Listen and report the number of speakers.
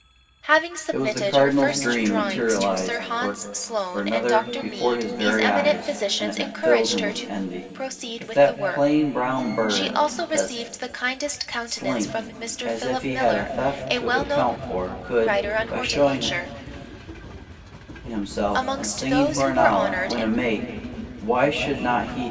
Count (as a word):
two